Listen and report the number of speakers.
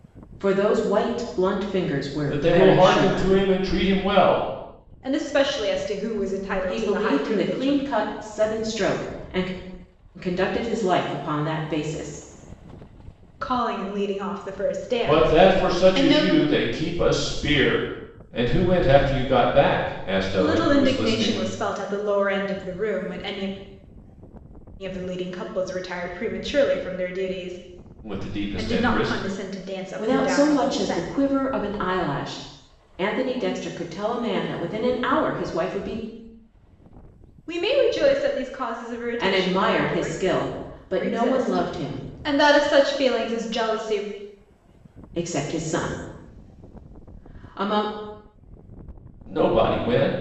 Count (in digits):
3